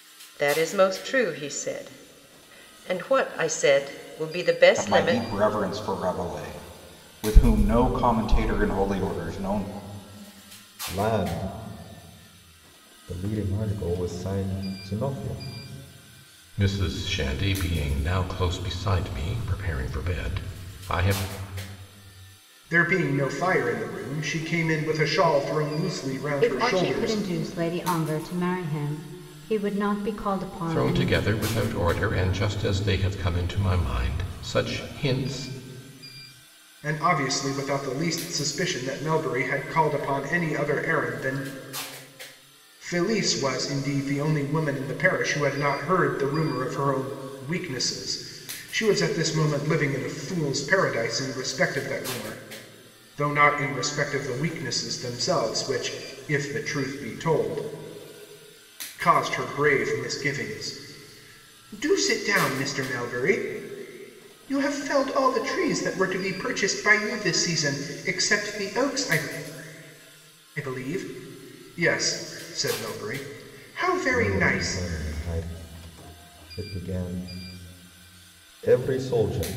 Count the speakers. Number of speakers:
six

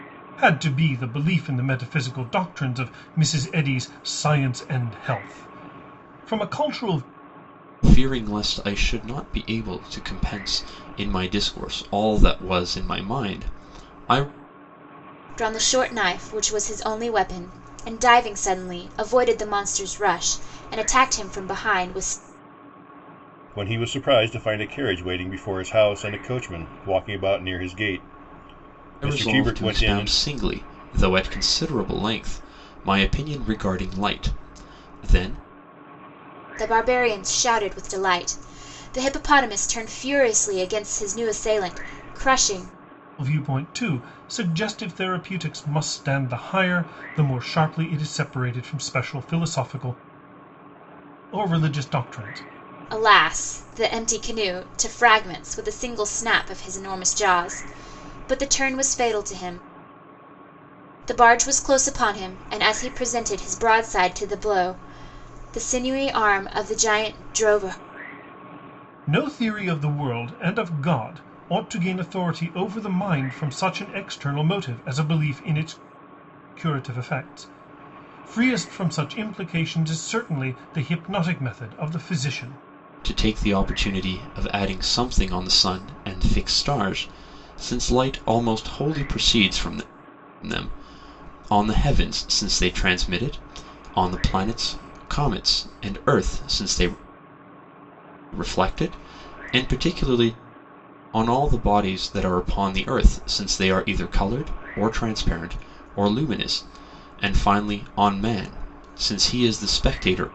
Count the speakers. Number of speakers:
four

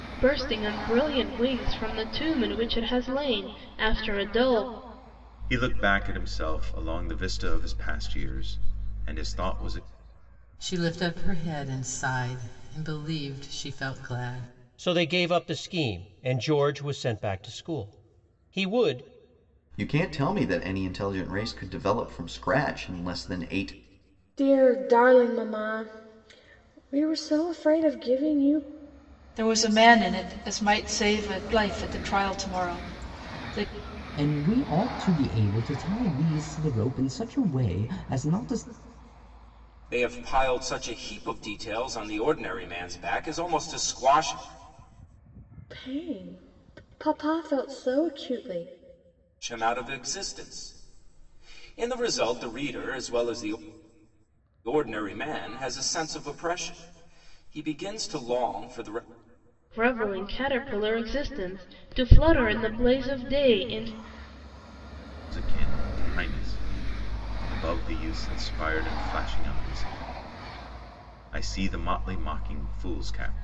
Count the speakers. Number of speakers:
nine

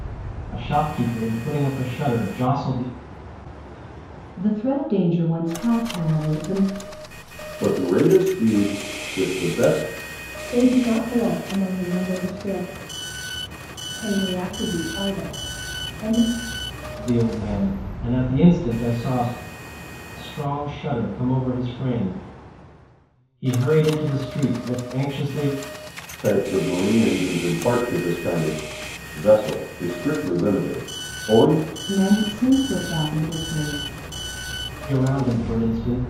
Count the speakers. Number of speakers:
four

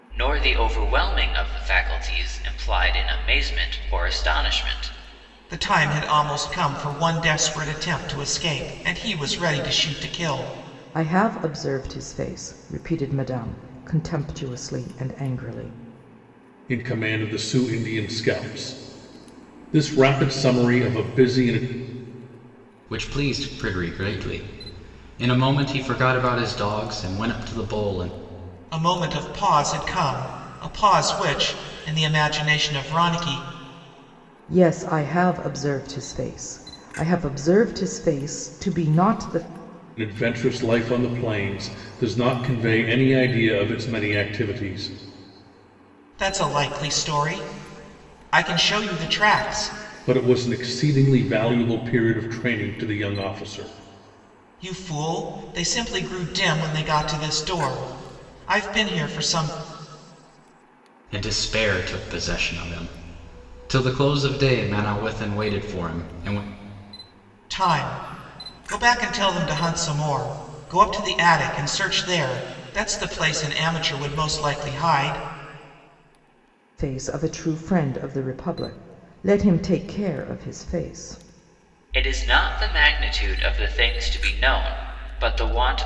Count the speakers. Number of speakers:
five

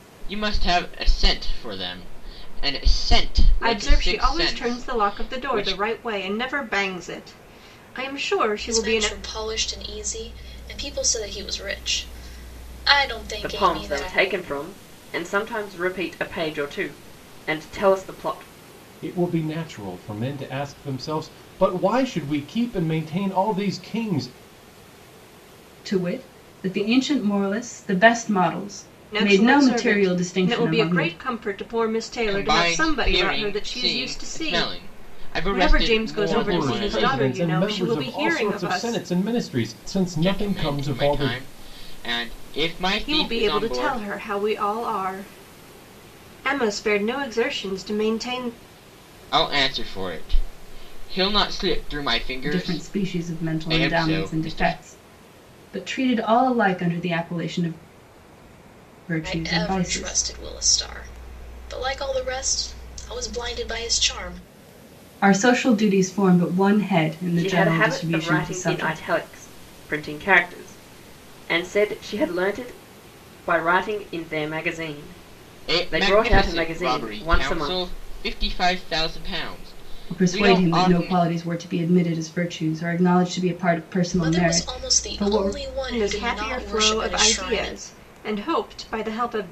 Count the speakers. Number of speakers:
six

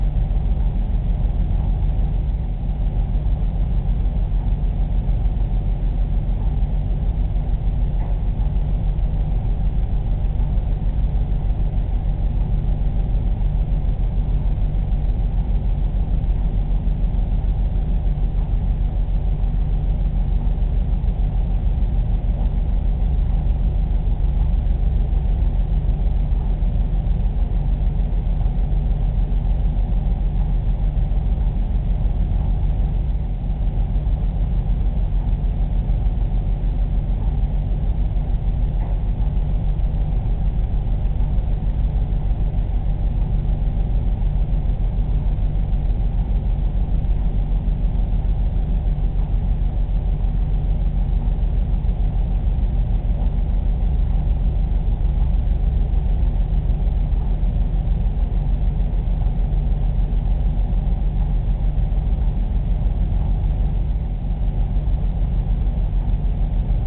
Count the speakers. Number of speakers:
zero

